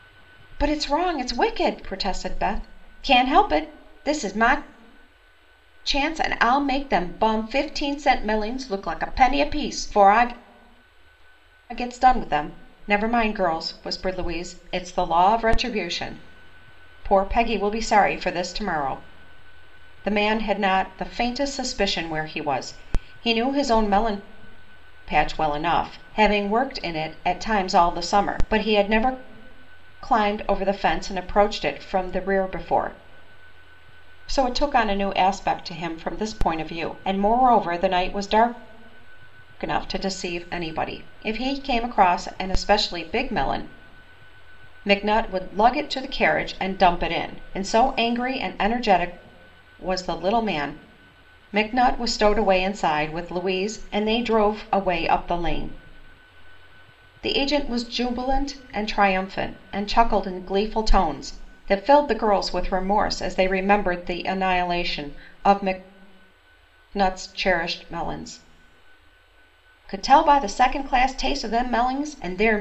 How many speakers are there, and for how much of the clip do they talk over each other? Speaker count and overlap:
one, no overlap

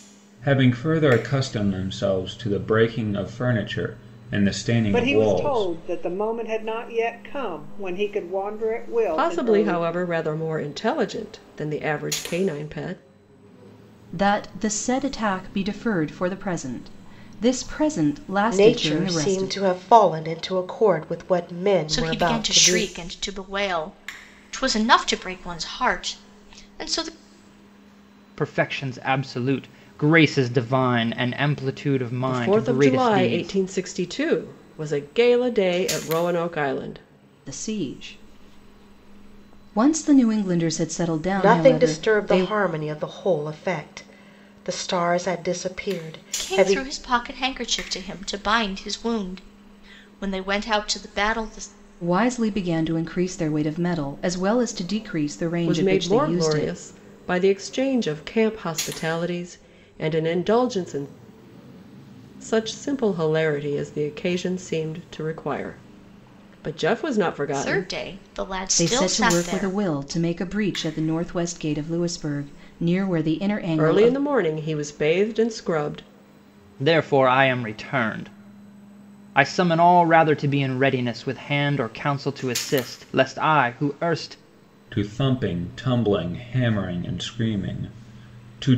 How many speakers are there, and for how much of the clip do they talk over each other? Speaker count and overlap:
seven, about 11%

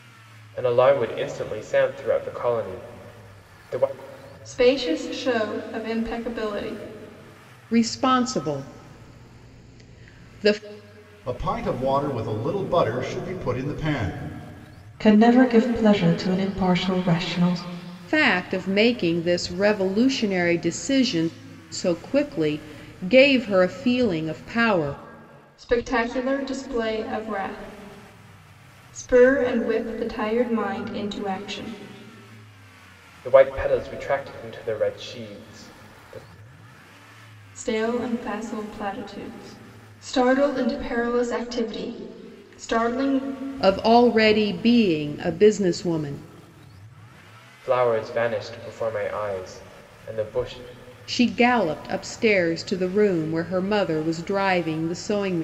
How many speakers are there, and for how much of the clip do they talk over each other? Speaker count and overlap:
five, no overlap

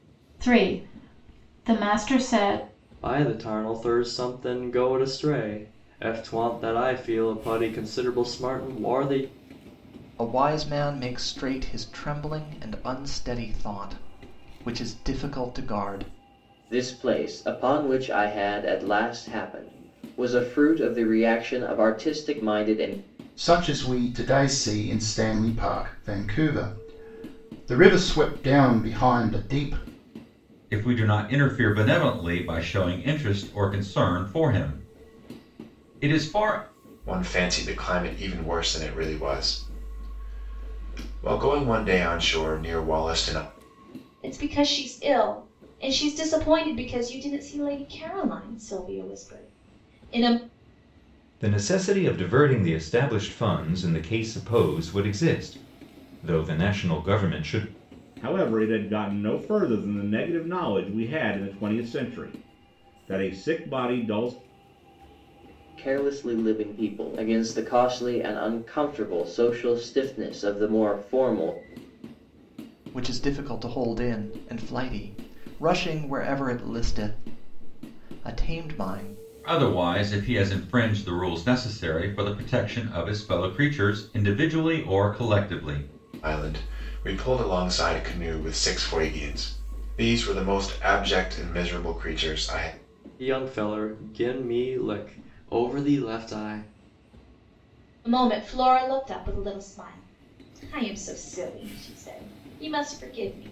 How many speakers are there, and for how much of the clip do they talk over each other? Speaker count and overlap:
ten, no overlap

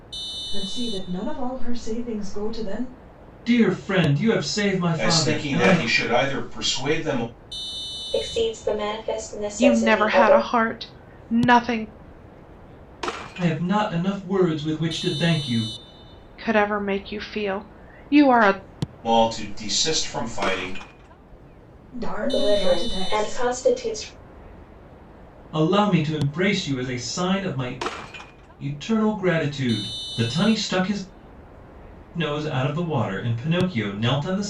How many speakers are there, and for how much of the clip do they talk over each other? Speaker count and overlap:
five, about 9%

